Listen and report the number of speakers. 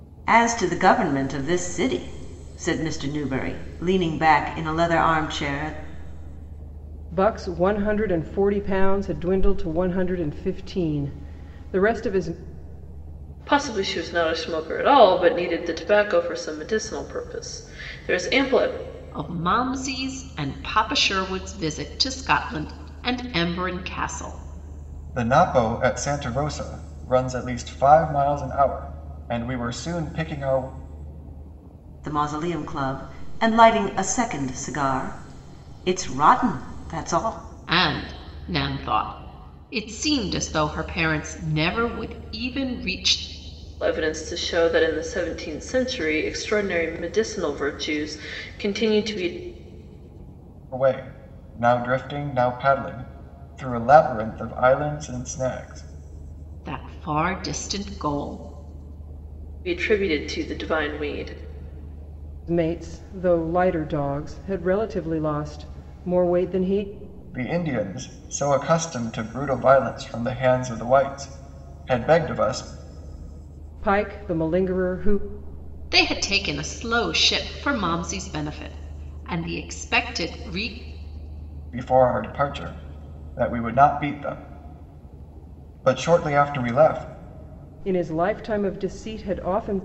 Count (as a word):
five